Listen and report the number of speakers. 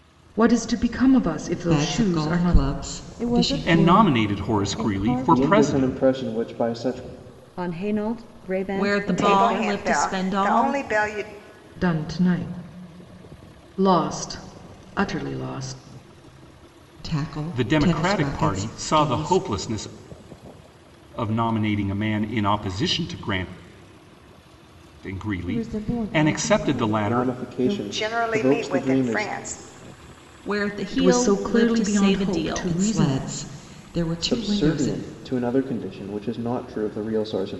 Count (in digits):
8